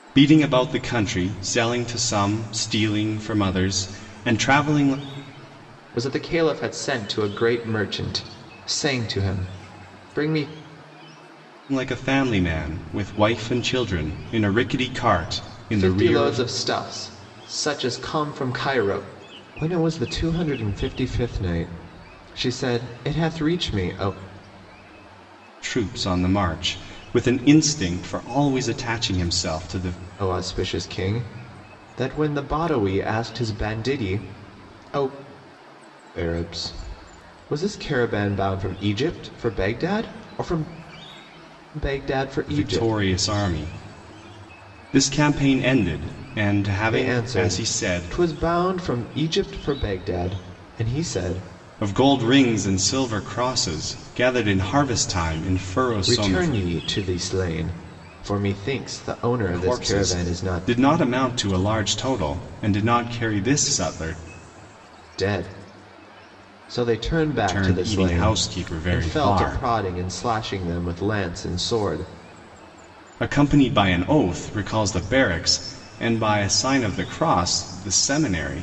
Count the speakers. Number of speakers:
2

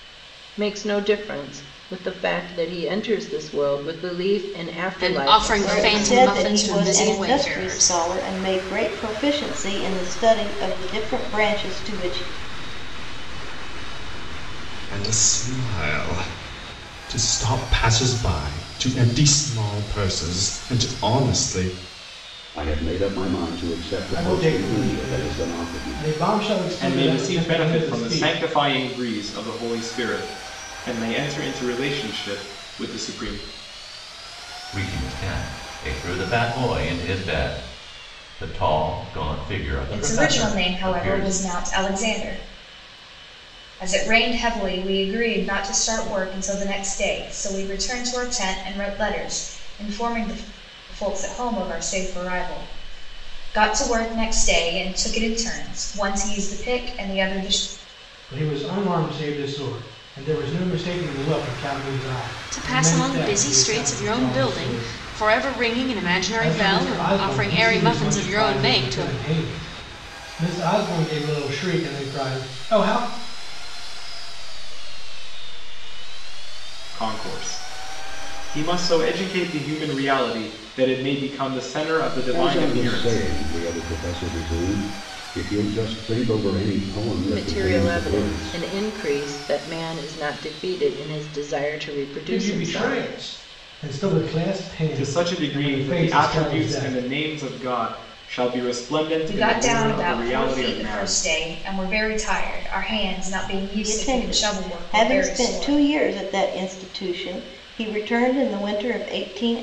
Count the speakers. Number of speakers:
10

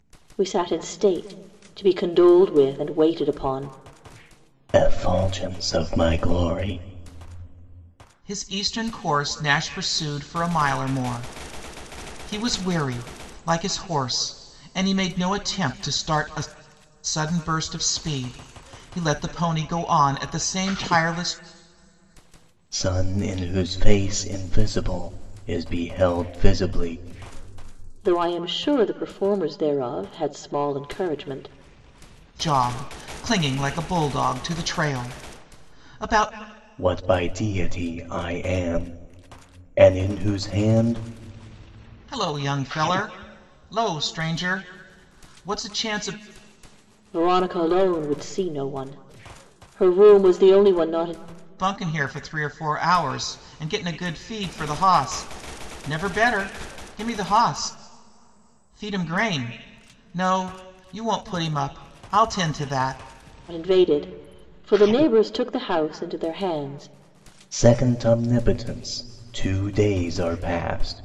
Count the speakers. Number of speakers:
3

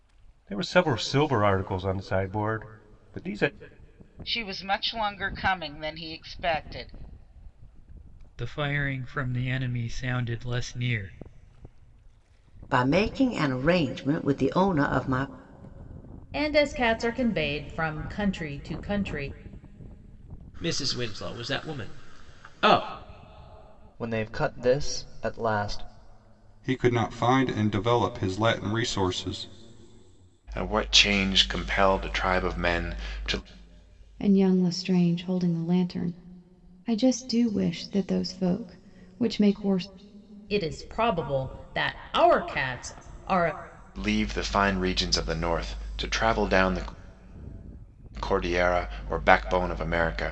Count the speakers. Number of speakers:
10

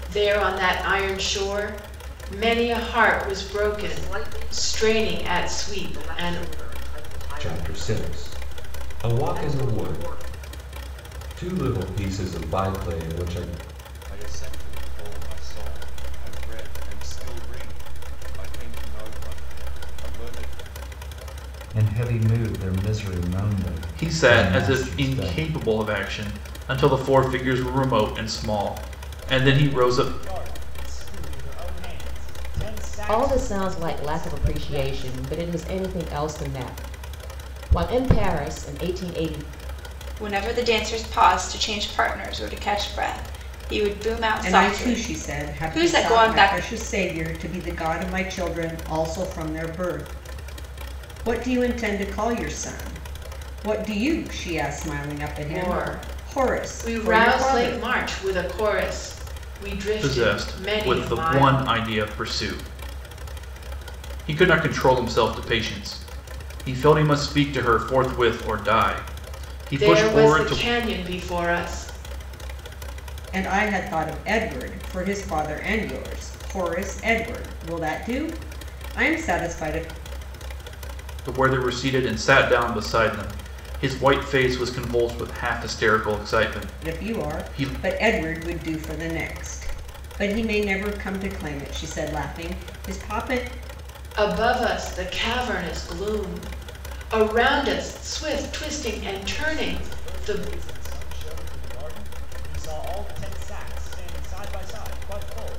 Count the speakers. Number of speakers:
10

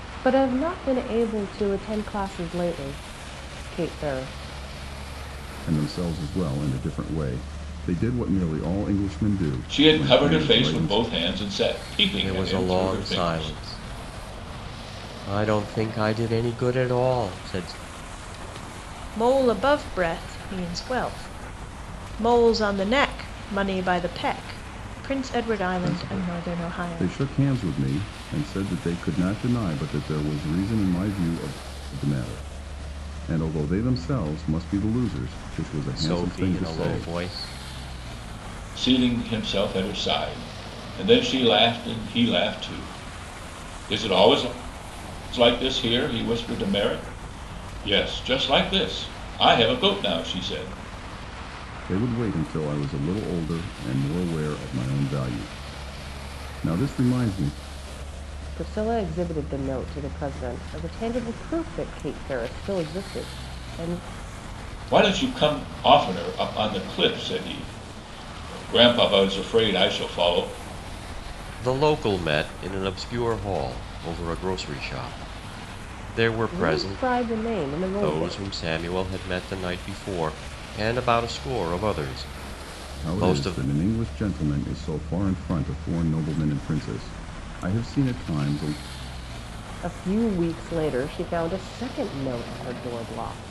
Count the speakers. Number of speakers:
5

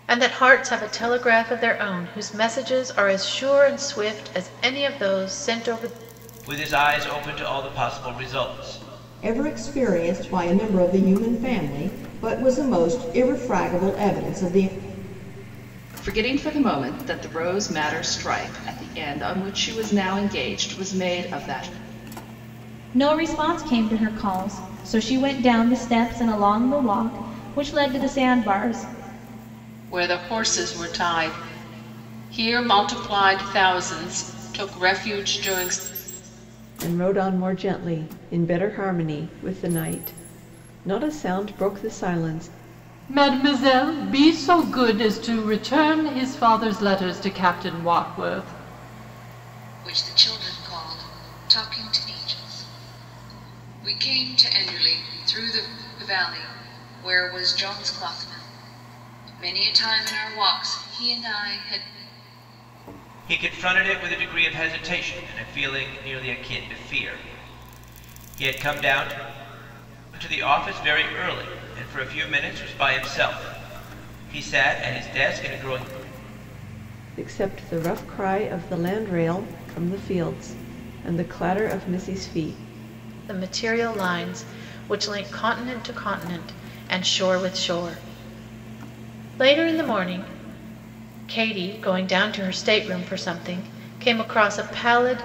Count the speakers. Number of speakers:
9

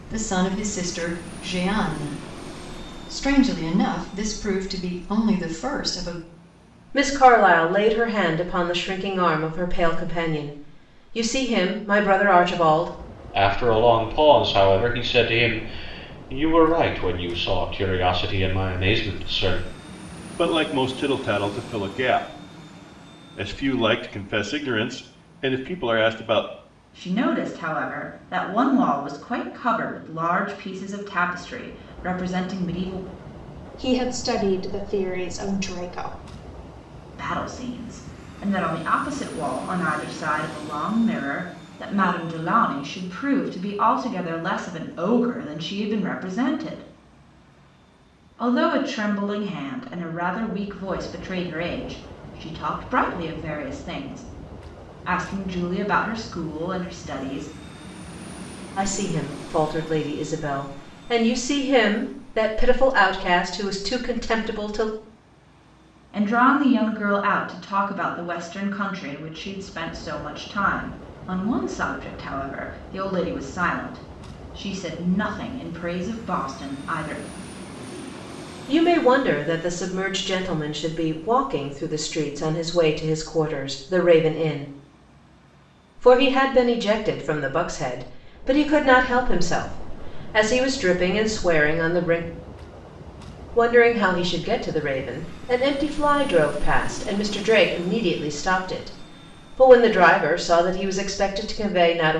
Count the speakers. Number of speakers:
6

